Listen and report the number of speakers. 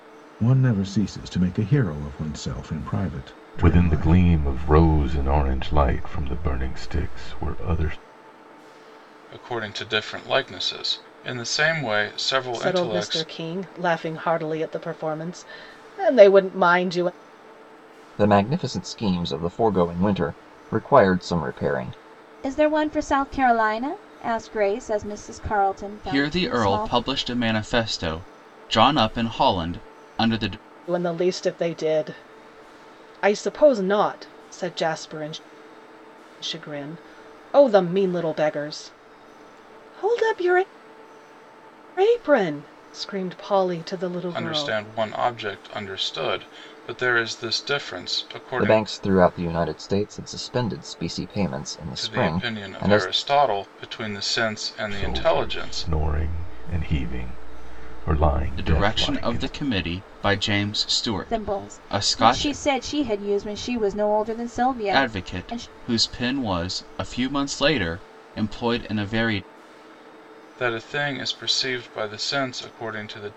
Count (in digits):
7